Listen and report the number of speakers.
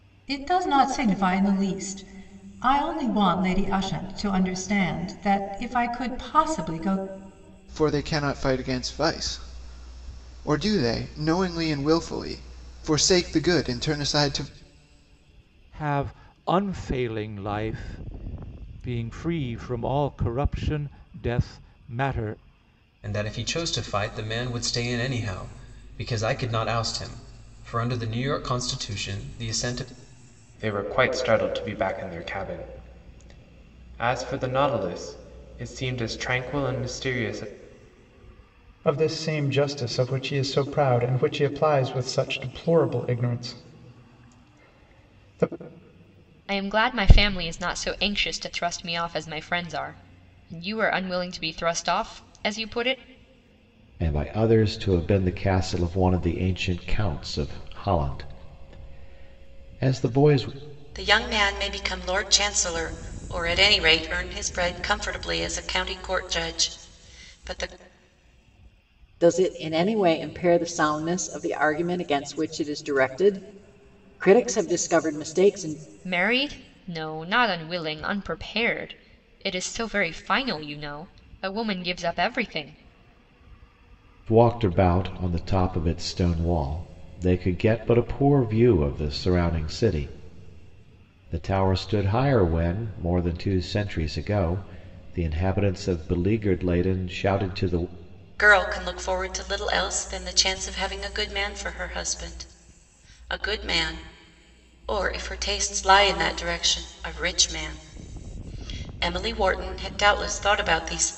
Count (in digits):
10